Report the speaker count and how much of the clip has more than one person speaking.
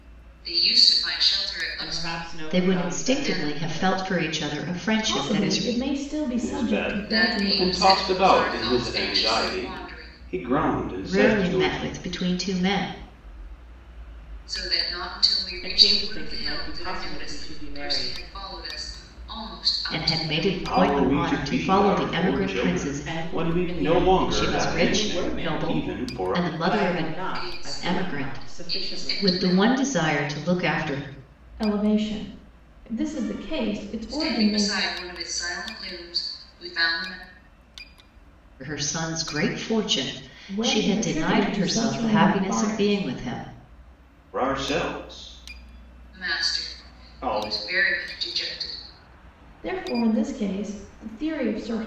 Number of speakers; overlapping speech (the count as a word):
five, about 47%